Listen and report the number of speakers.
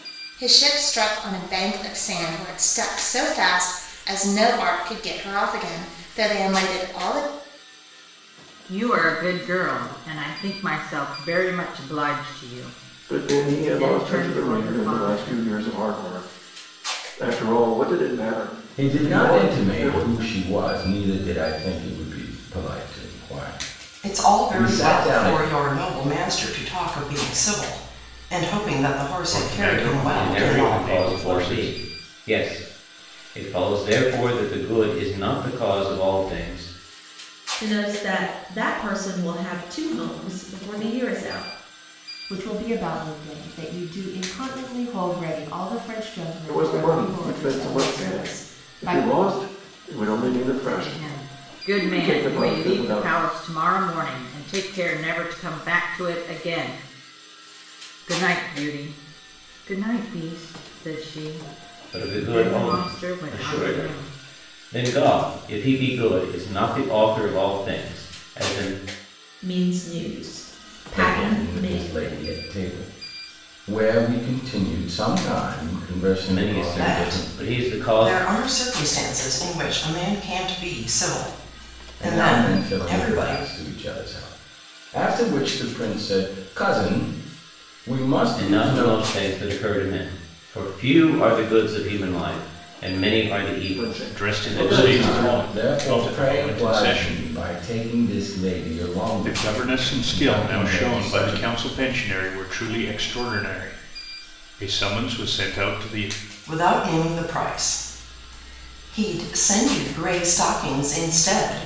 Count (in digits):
9